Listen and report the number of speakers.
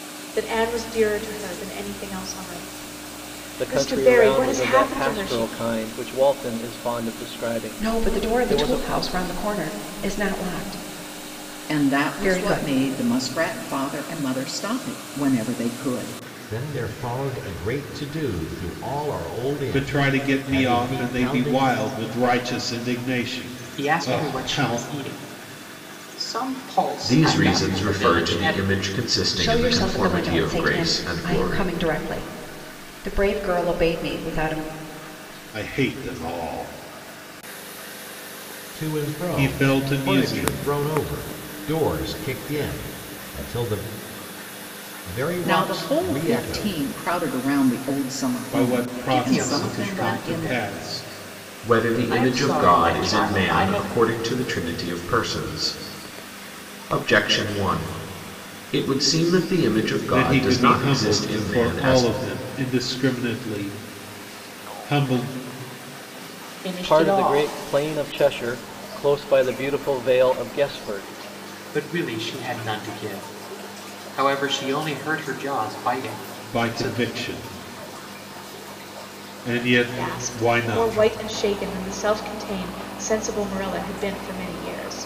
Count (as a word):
eight